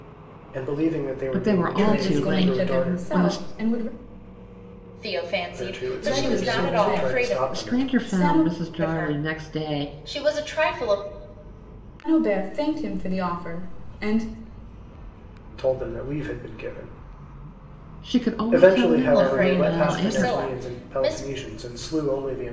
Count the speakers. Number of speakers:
four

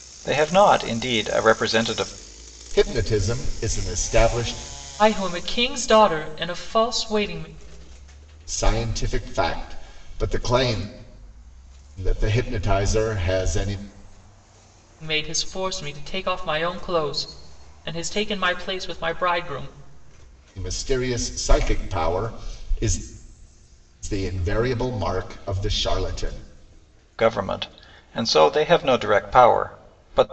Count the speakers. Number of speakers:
three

